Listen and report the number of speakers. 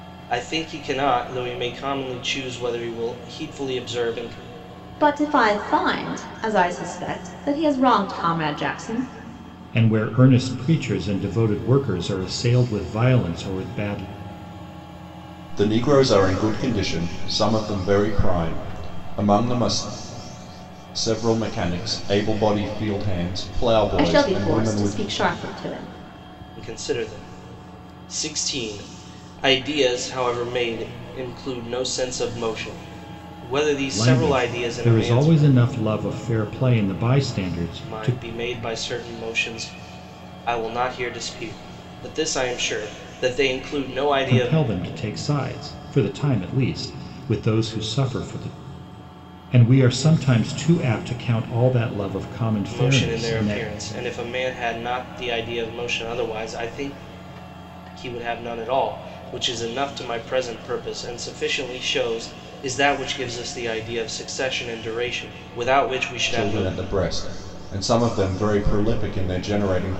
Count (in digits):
4